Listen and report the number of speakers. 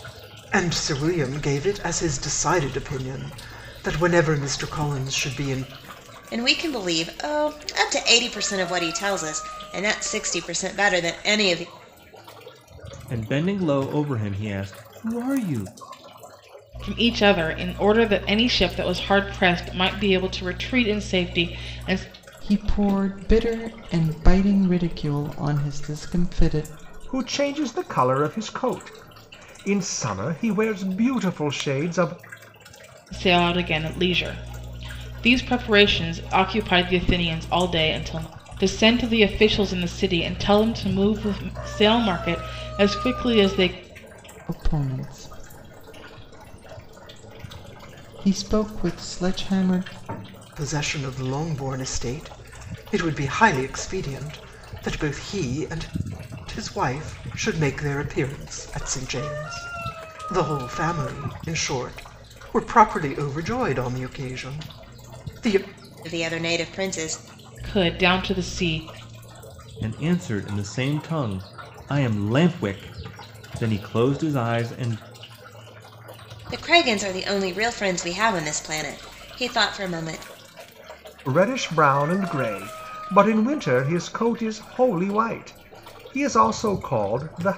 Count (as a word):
six